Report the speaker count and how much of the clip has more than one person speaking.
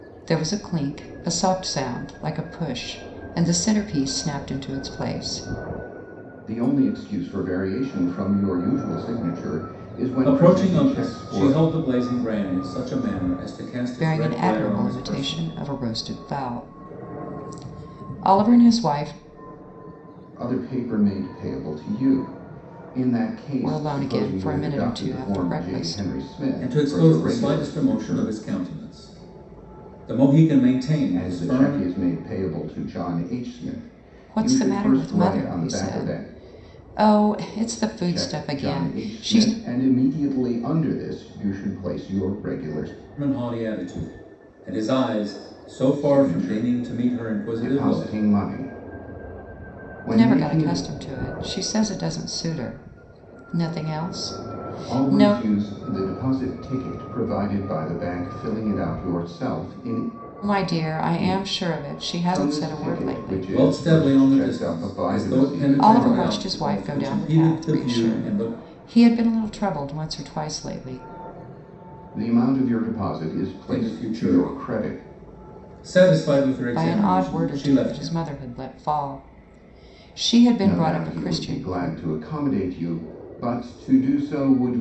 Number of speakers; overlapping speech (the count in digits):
3, about 31%